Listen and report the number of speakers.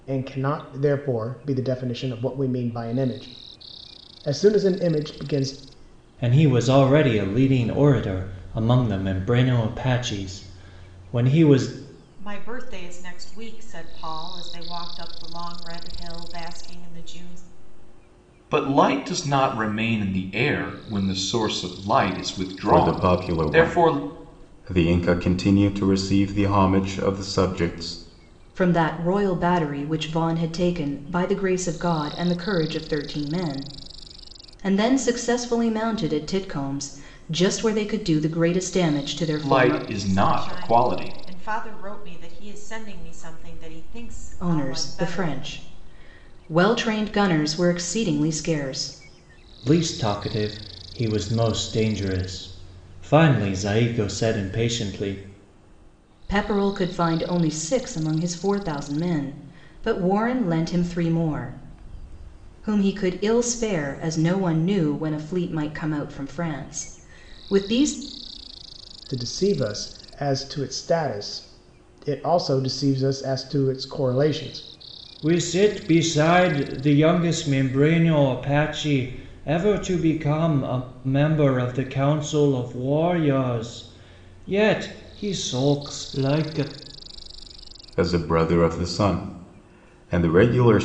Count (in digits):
6